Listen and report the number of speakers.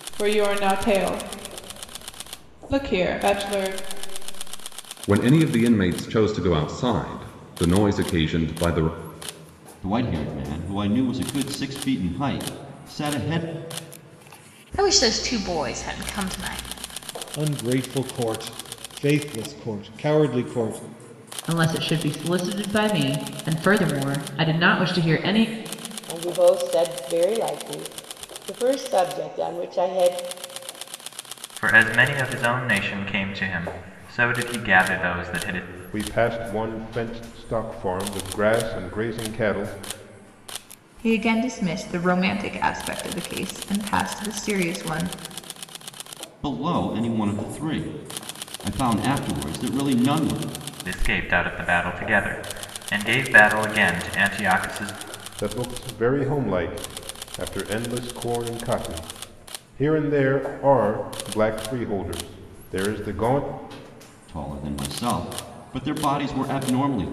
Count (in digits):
10